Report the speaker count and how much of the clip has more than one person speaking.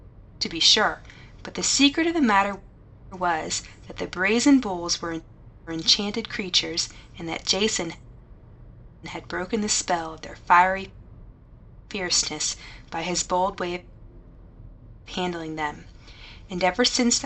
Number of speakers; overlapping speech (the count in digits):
1, no overlap